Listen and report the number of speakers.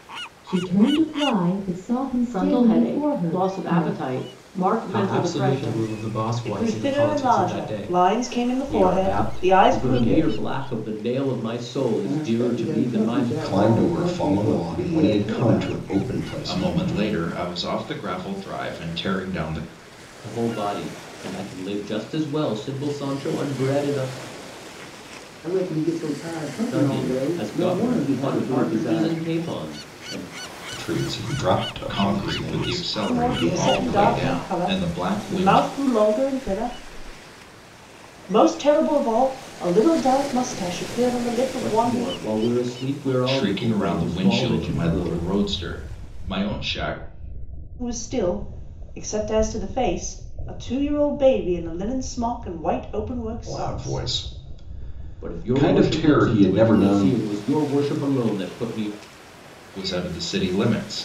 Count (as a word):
nine